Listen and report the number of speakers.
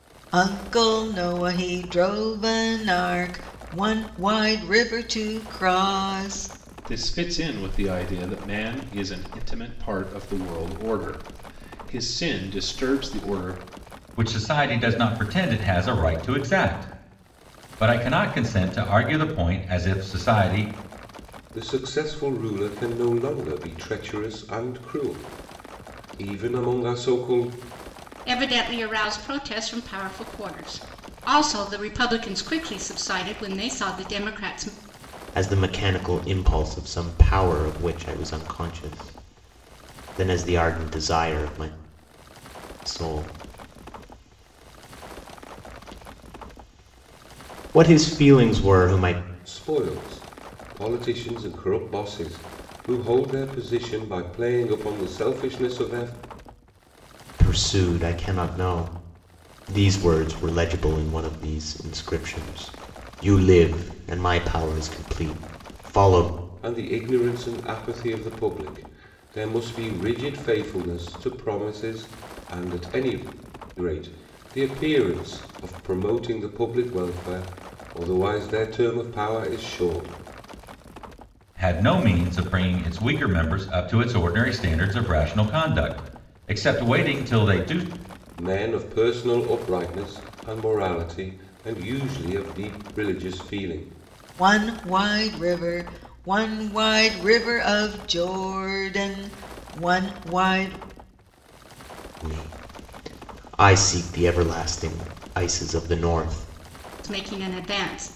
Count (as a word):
six